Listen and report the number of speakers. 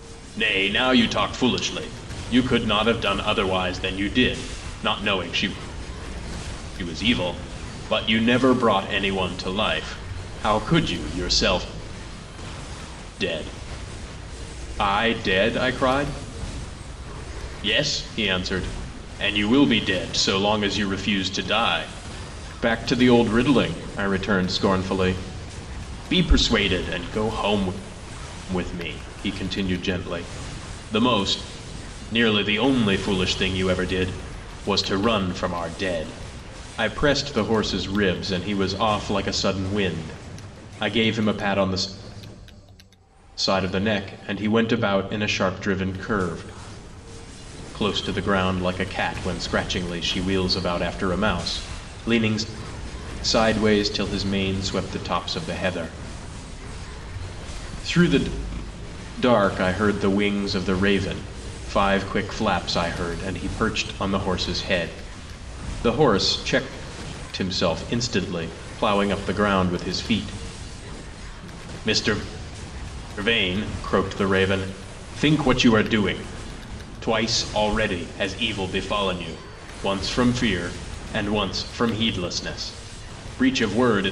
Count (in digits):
1